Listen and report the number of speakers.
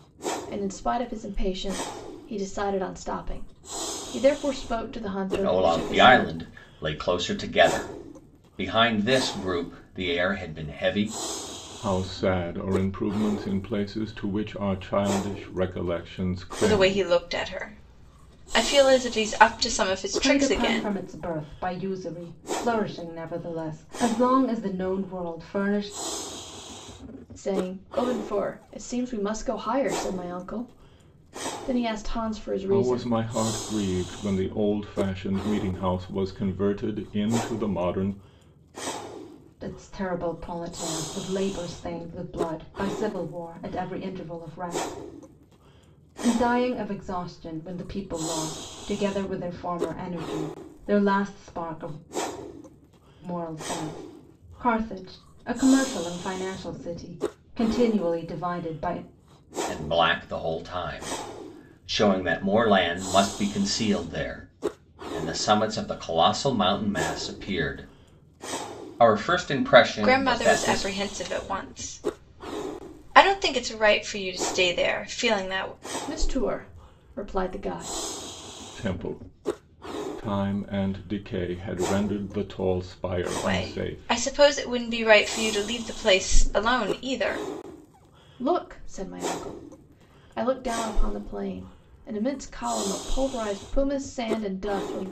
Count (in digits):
5